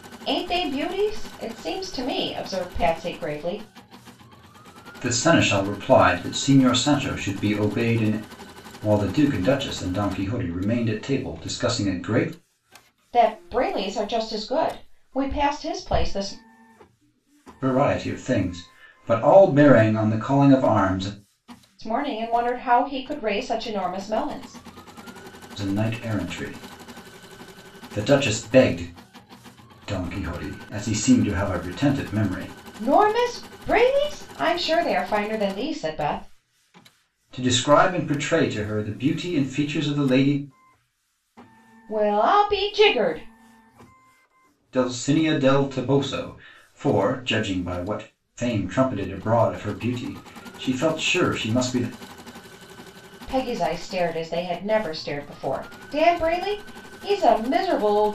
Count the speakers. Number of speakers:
2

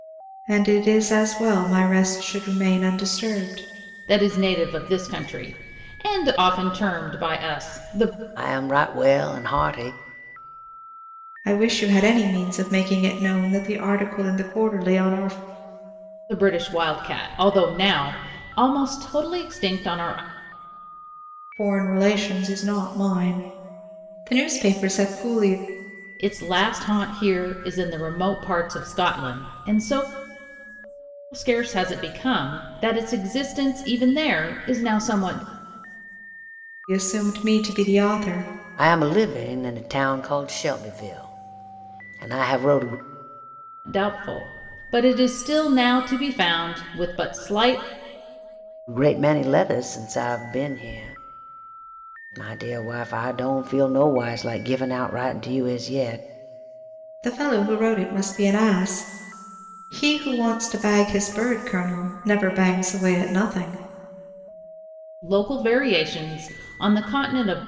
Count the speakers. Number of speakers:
3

